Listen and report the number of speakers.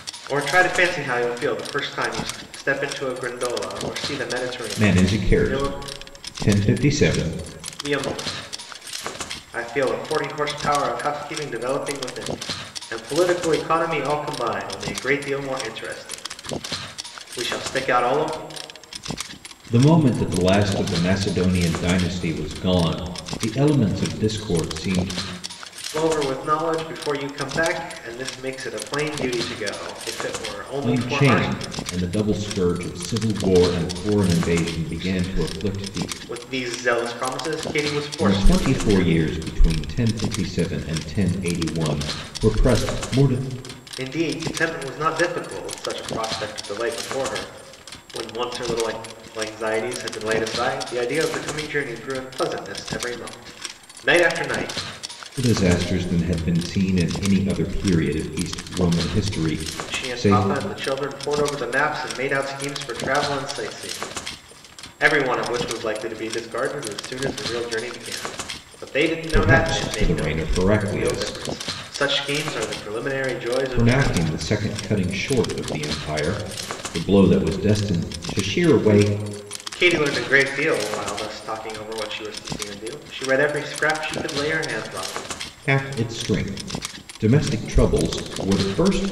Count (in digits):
2